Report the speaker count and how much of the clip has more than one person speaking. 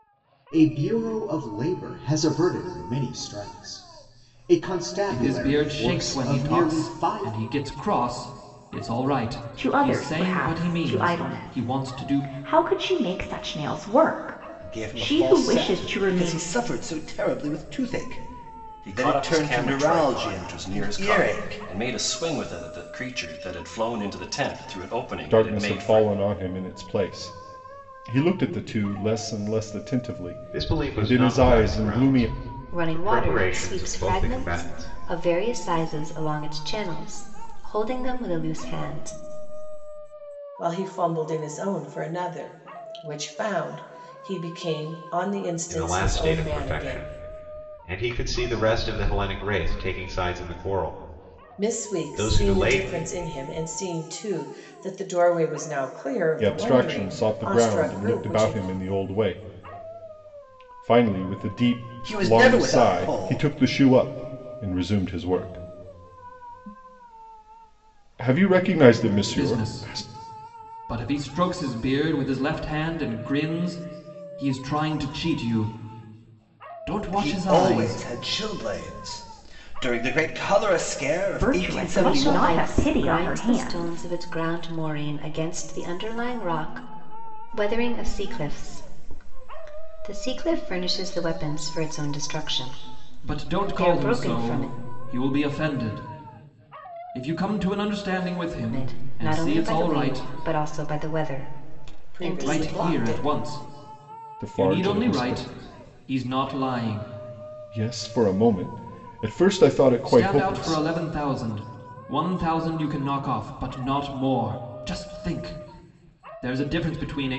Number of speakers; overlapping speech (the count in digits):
9, about 29%